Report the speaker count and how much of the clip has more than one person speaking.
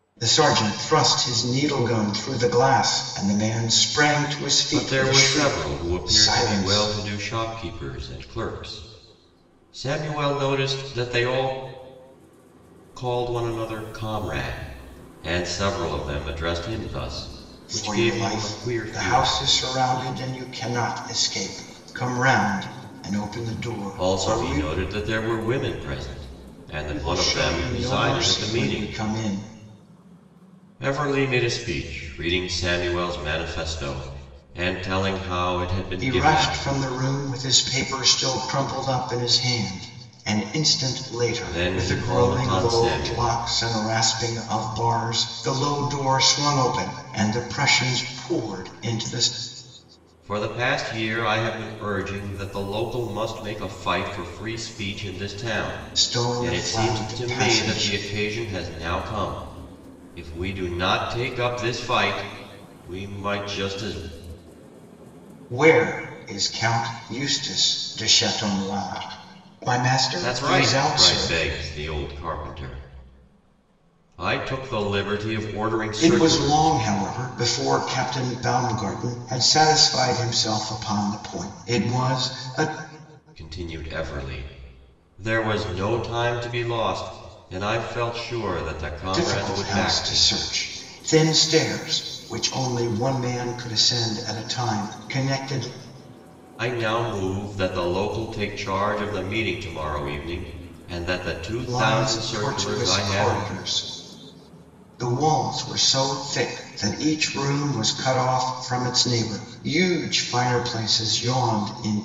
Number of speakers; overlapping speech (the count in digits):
2, about 15%